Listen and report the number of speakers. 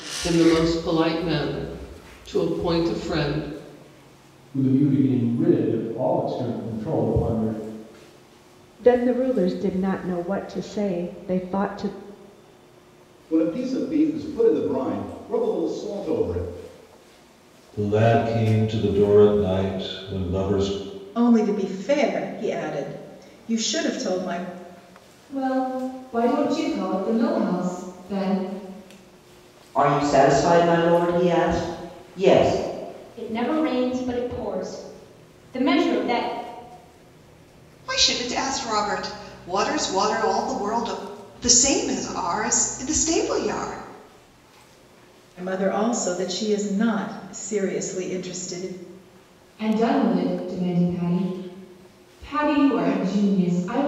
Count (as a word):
ten